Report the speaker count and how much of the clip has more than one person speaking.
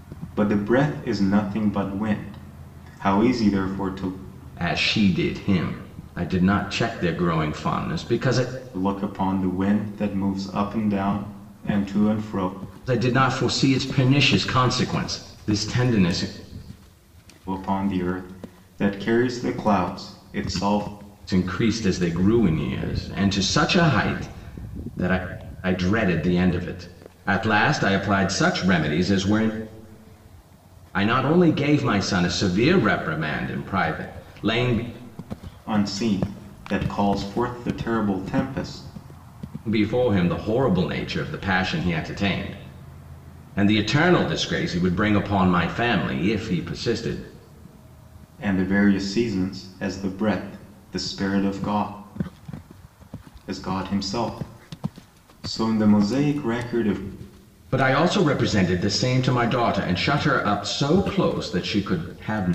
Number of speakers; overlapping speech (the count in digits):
2, no overlap